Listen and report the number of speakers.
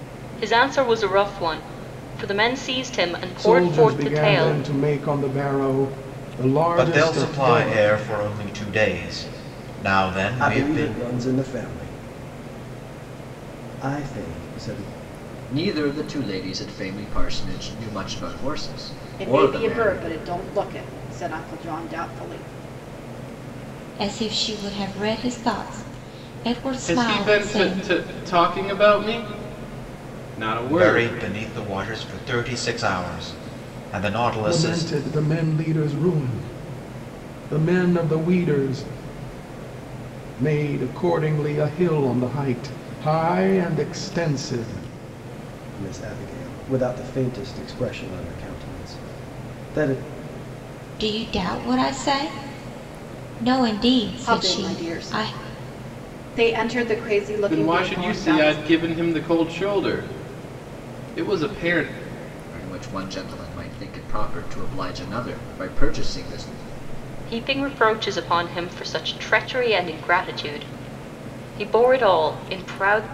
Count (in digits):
8